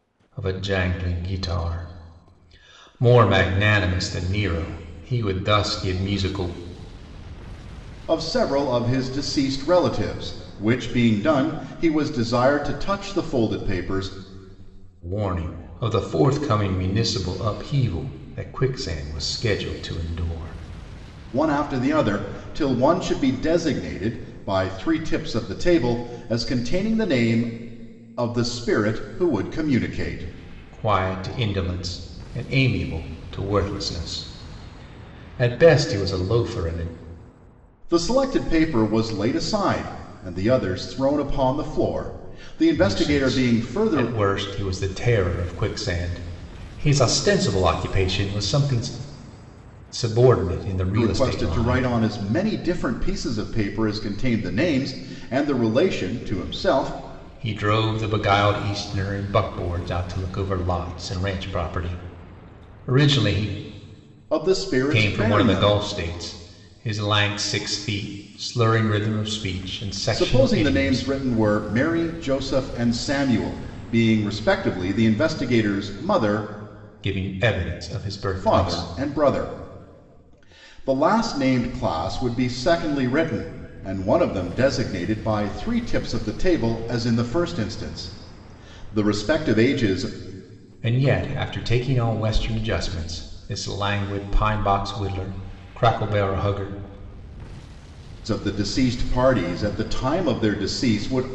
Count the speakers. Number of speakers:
two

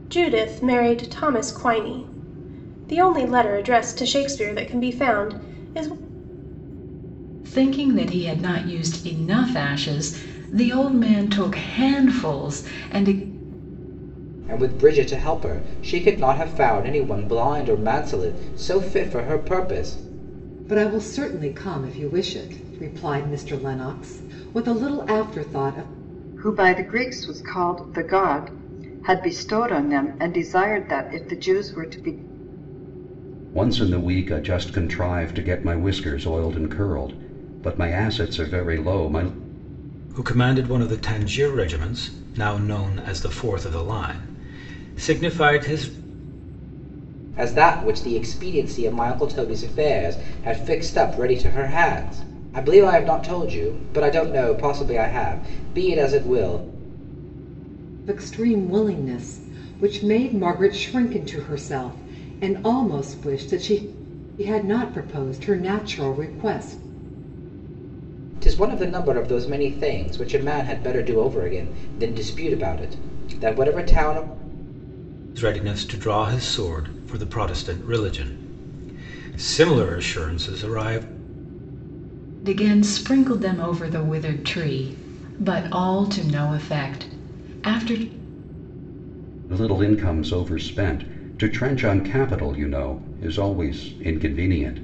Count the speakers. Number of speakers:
seven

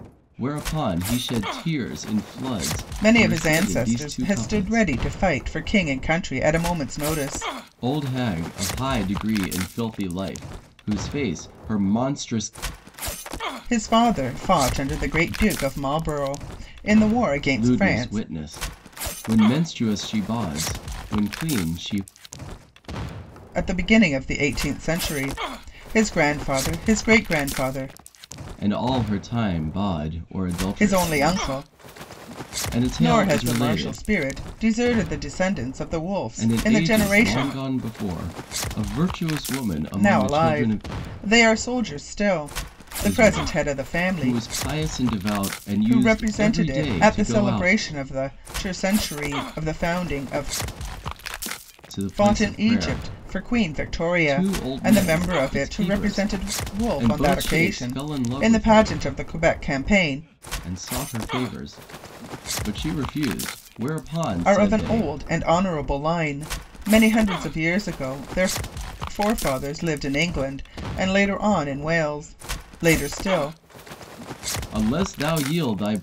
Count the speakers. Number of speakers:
two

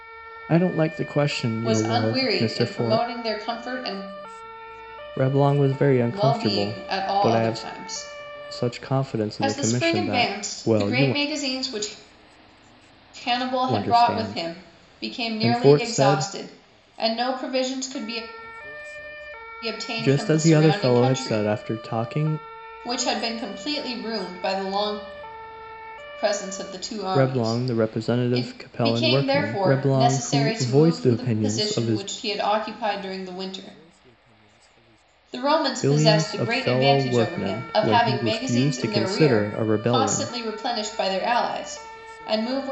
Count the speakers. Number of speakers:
two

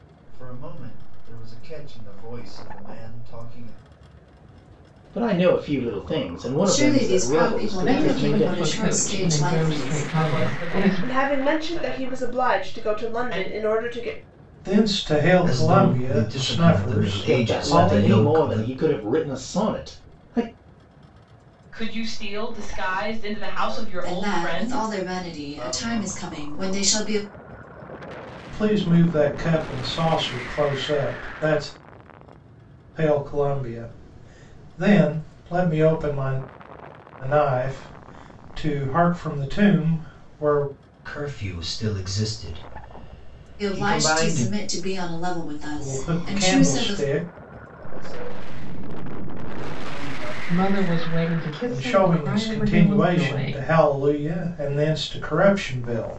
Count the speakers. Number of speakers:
eight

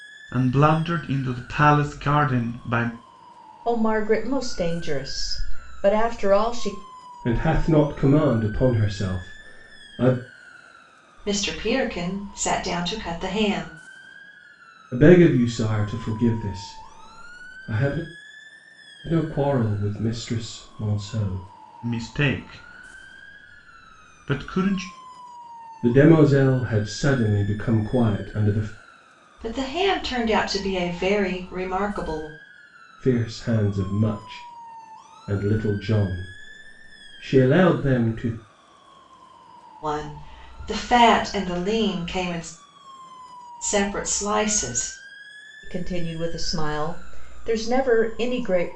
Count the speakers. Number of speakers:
four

